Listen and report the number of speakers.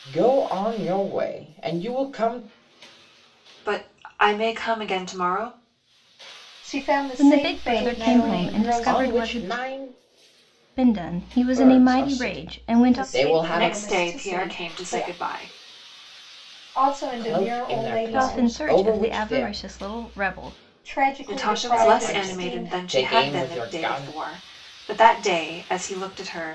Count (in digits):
4